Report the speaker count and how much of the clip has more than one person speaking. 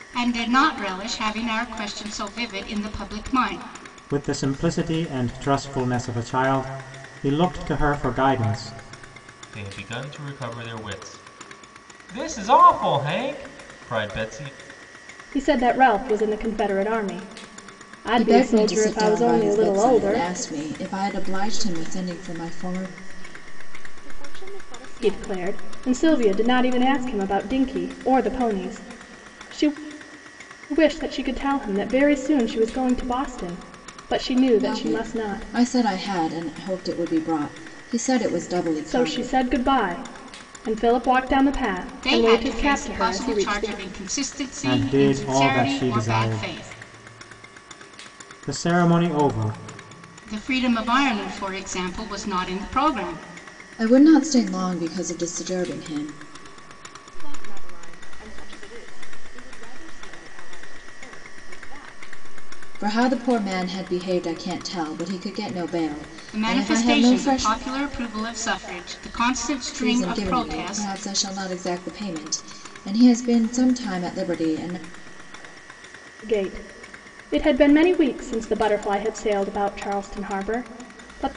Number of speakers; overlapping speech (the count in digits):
6, about 16%